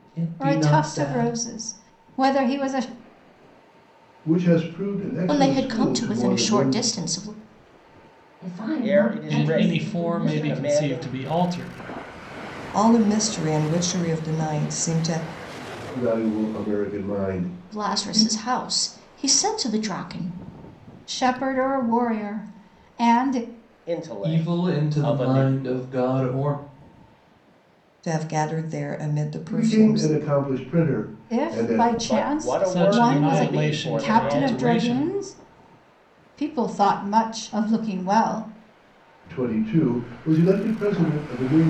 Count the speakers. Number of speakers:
8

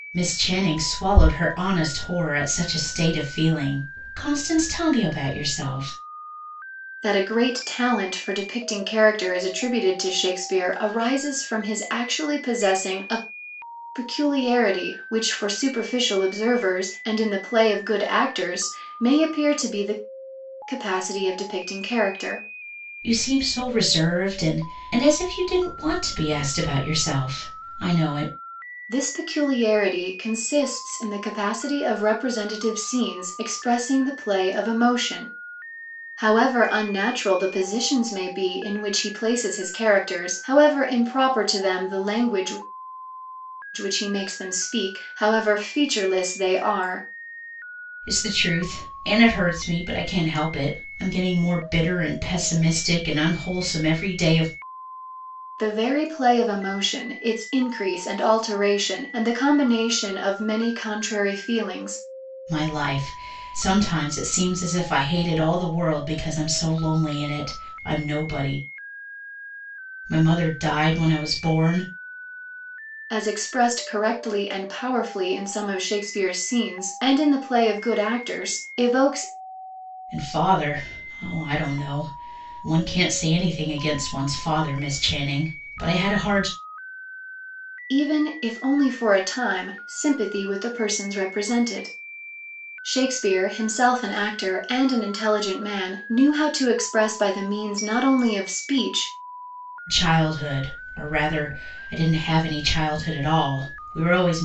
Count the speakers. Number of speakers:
2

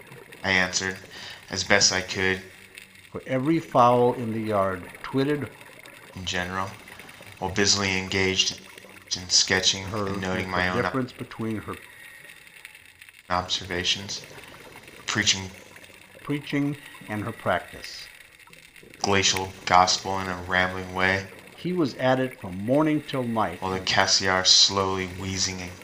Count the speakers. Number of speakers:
2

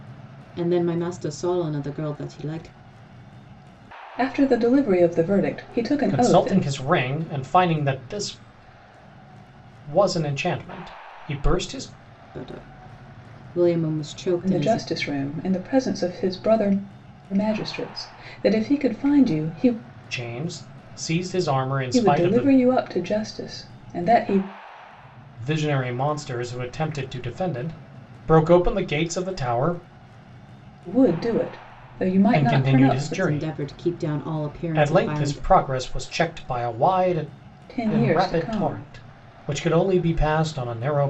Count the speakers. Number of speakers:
3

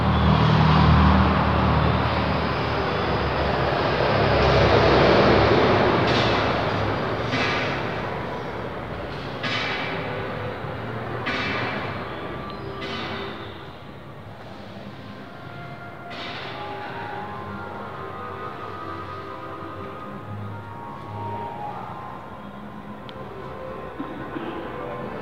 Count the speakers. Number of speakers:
0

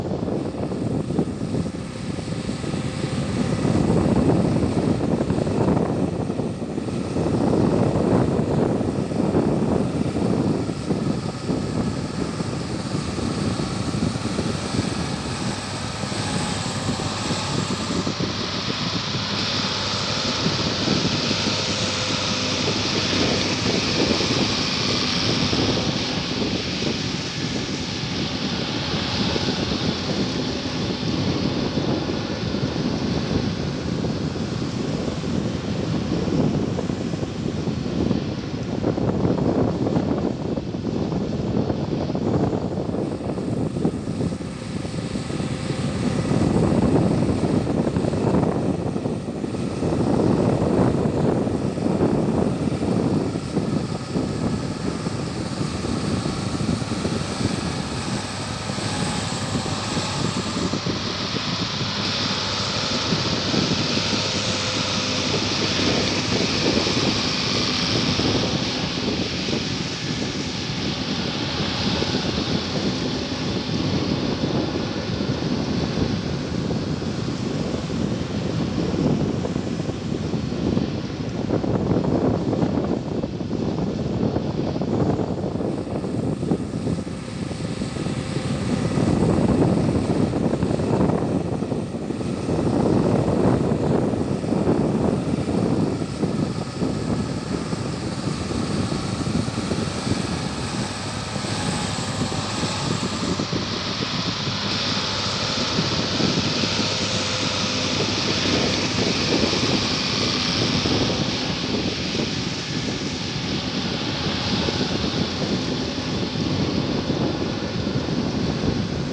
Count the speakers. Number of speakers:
0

